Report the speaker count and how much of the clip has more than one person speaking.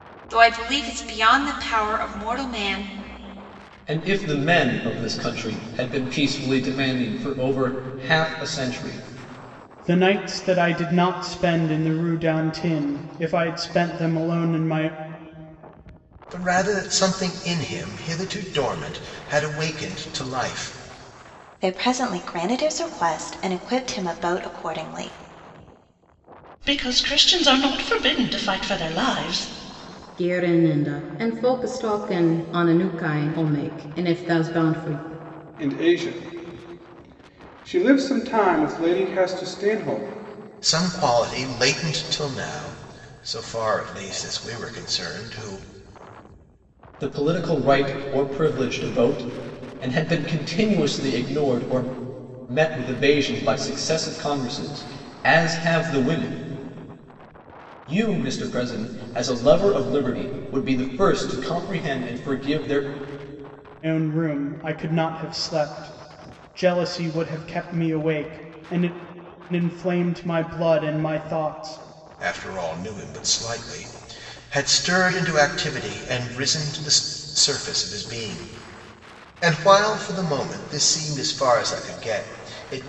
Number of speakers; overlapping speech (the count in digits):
8, no overlap